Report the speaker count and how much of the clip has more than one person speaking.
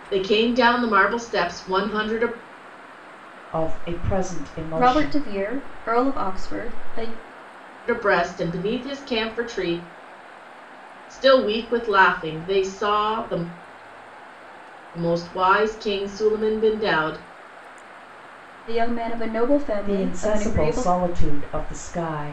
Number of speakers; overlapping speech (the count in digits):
3, about 8%